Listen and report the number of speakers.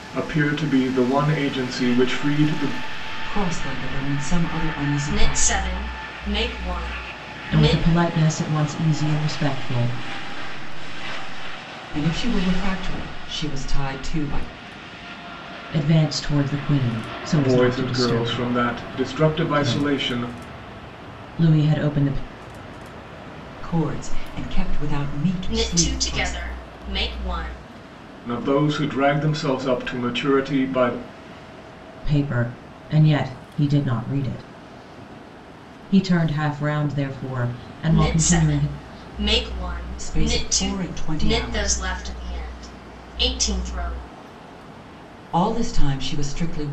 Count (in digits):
5